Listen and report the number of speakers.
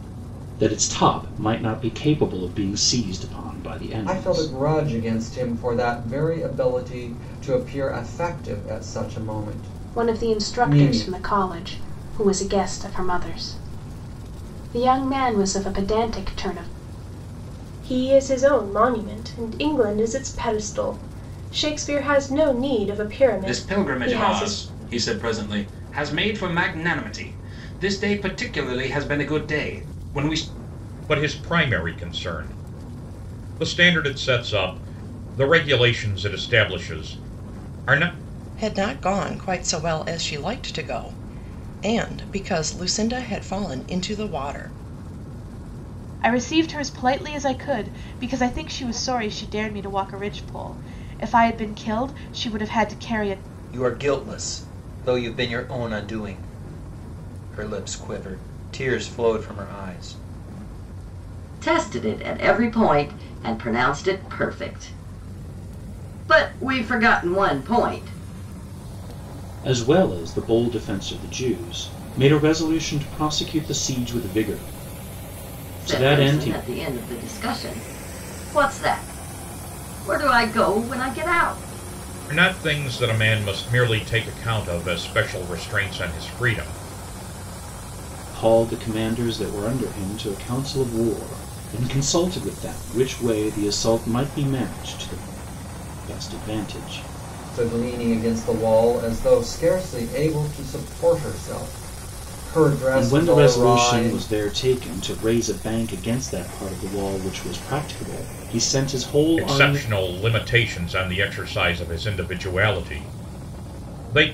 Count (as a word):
ten